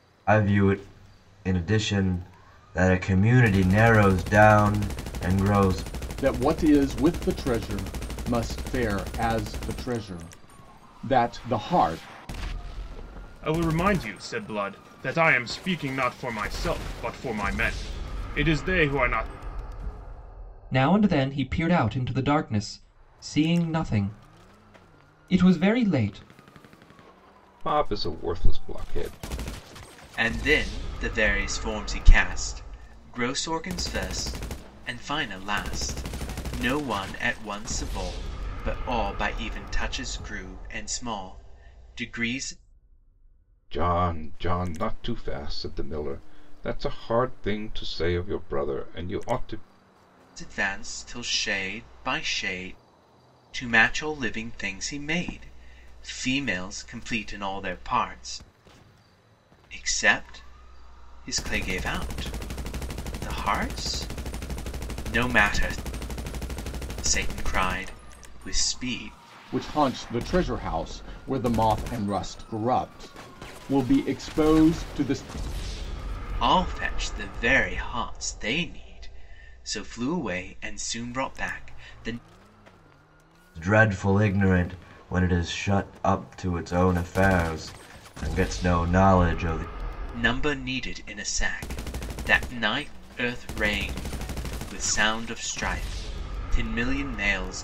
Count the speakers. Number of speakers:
6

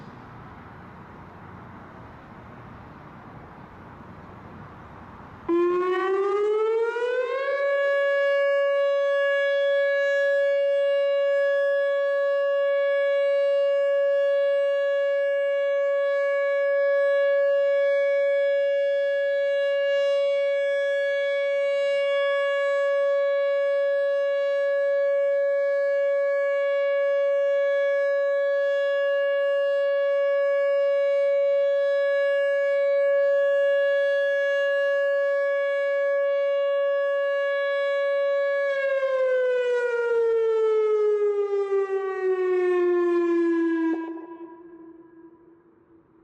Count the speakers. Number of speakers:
0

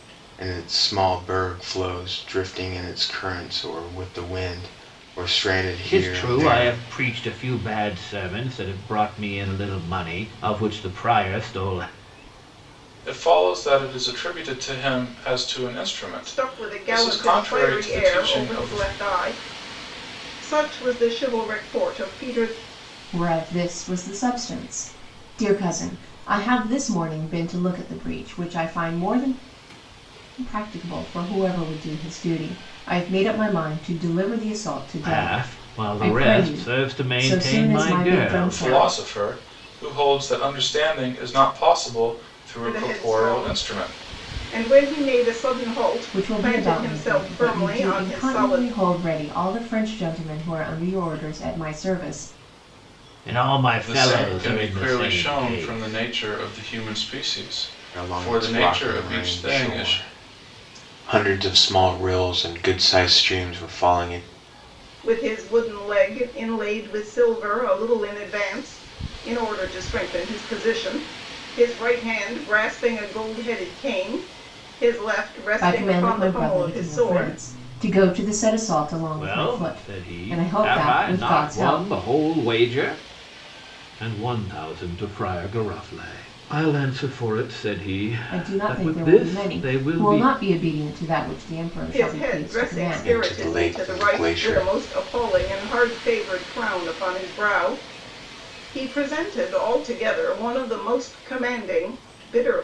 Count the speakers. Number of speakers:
5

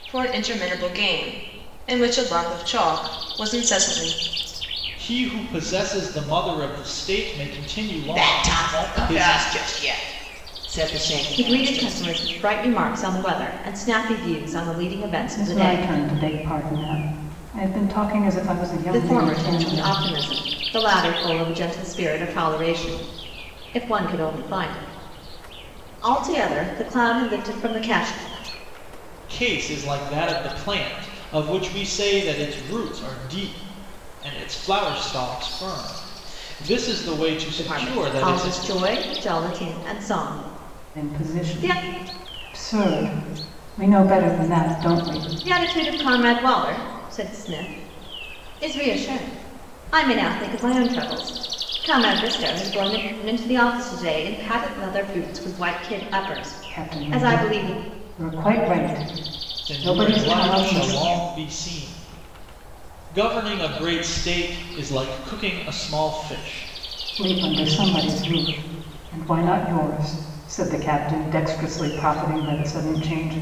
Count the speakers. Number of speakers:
5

